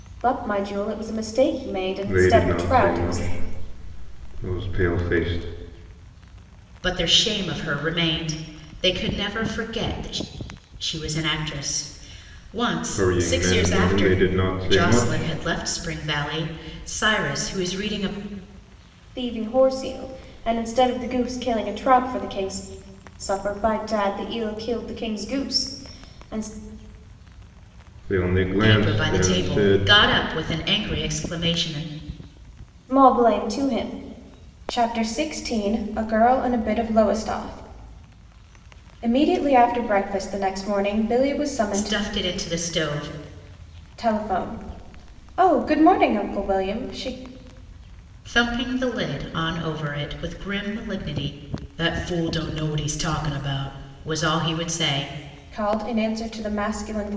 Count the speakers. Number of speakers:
3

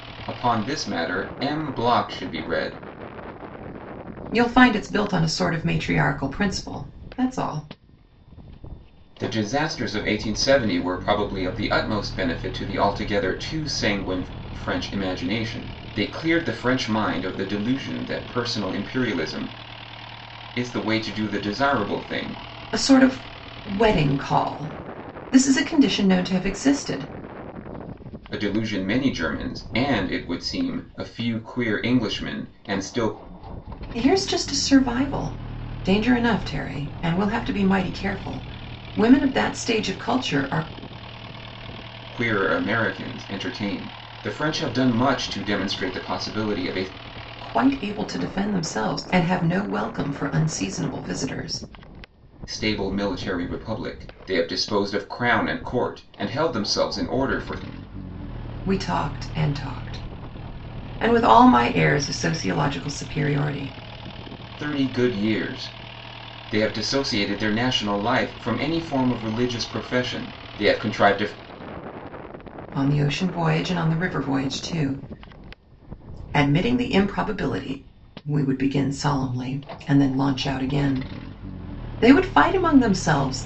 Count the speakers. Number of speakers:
2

